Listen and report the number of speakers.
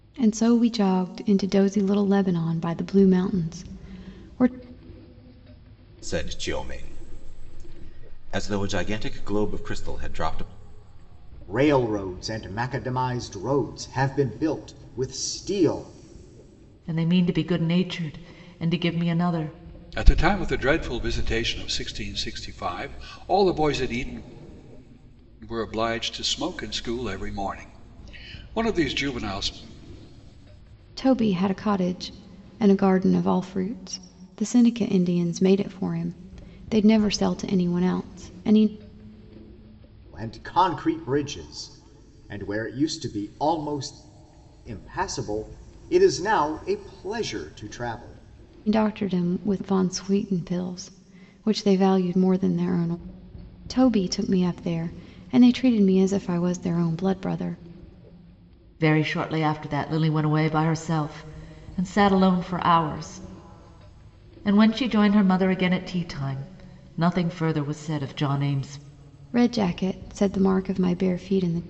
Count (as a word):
five